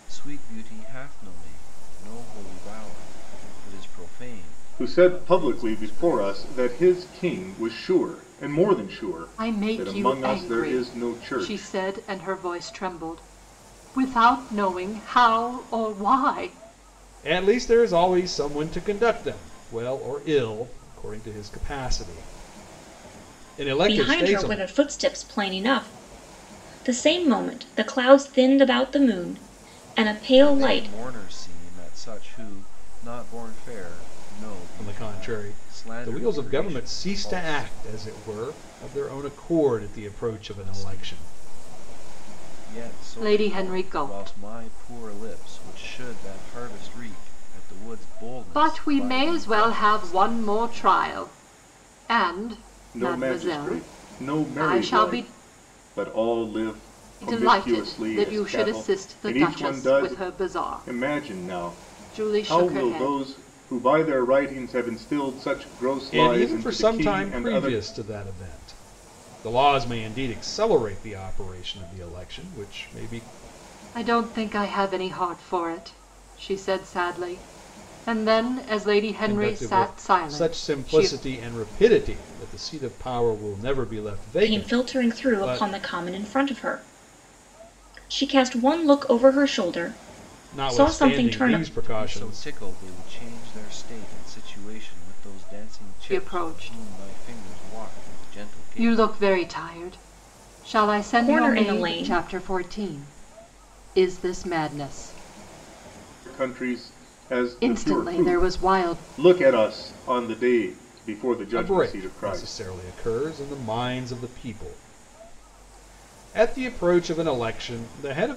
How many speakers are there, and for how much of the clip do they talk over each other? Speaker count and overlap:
5, about 30%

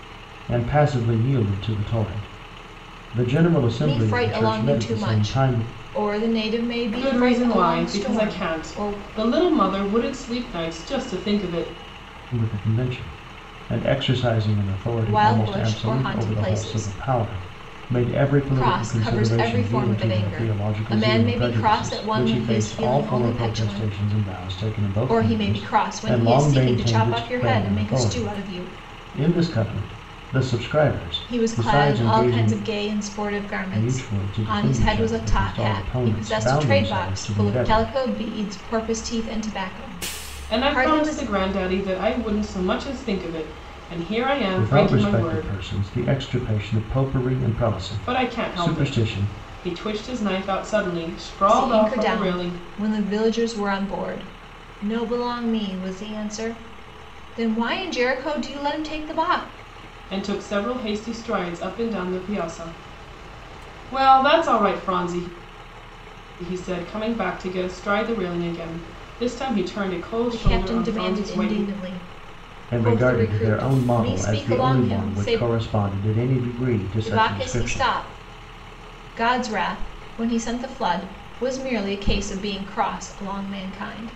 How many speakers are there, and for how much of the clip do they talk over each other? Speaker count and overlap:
3, about 37%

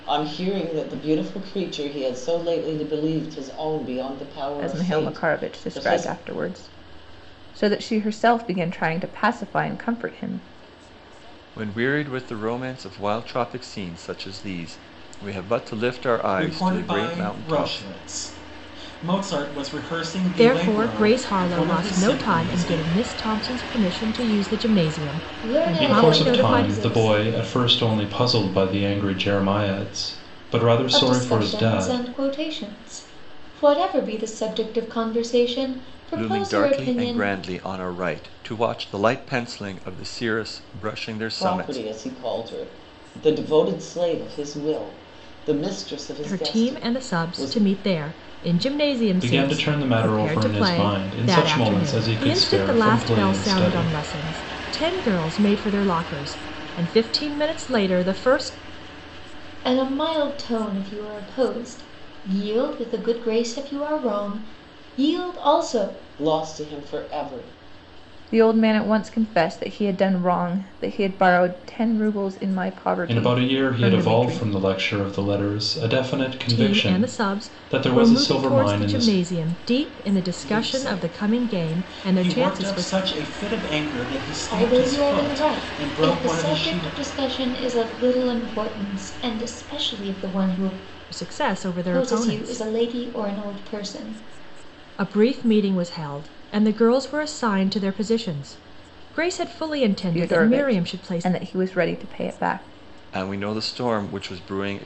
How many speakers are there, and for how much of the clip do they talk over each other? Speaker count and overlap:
7, about 26%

